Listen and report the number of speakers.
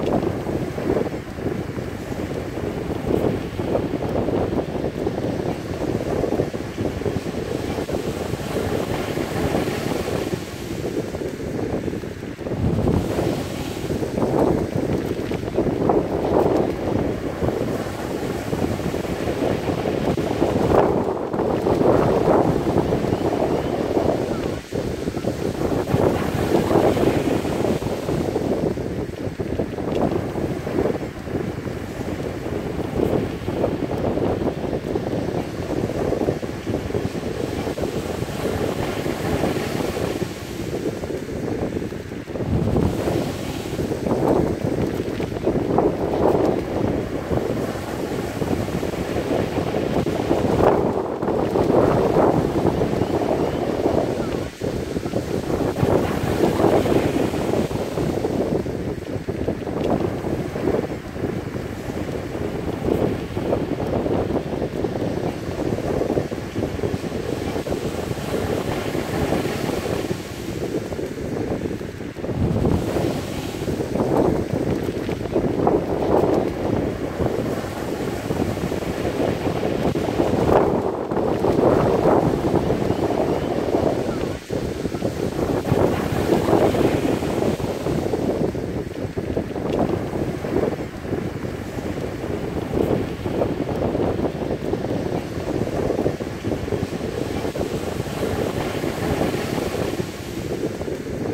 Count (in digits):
0